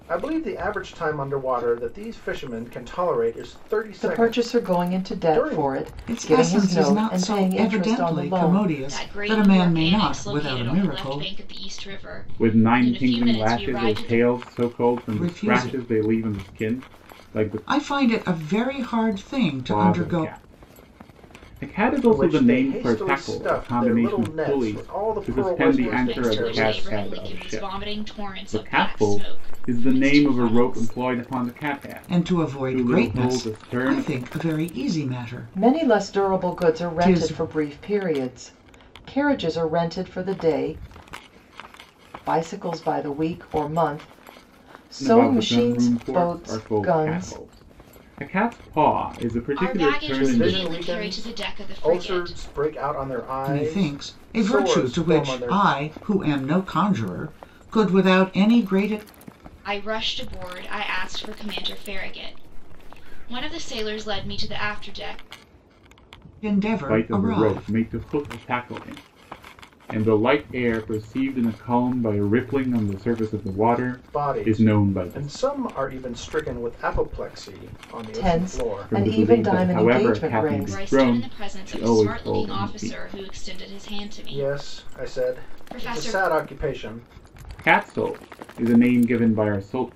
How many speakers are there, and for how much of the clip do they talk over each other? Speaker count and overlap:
5, about 45%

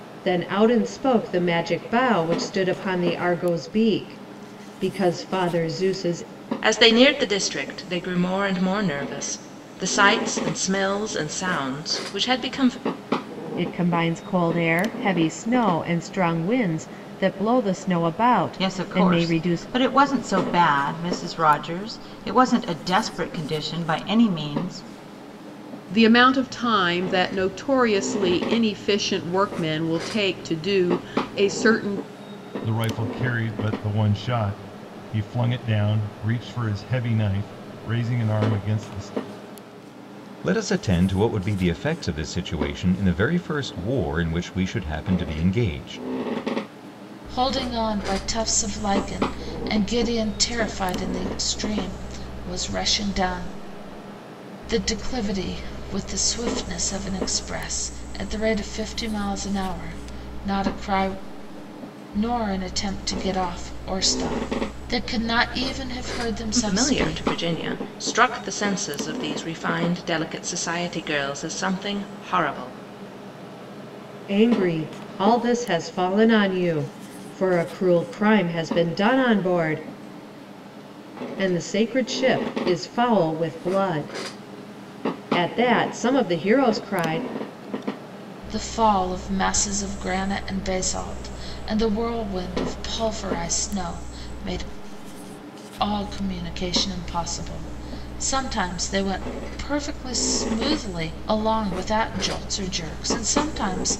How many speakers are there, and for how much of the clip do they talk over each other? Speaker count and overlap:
8, about 2%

